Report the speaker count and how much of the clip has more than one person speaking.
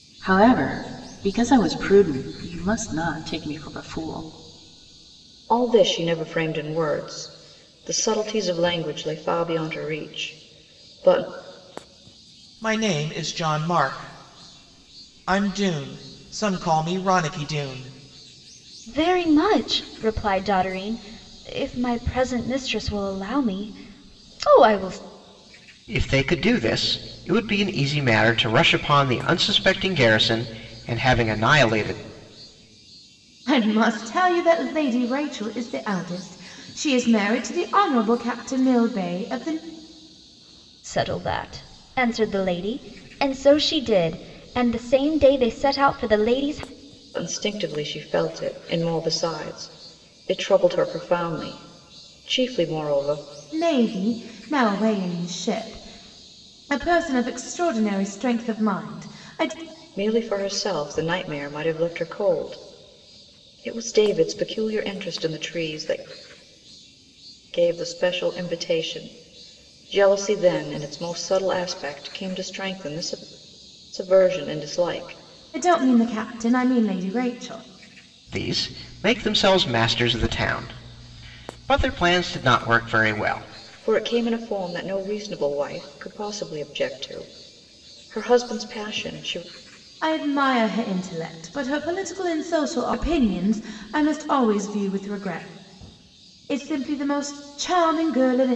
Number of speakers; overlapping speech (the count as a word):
six, no overlap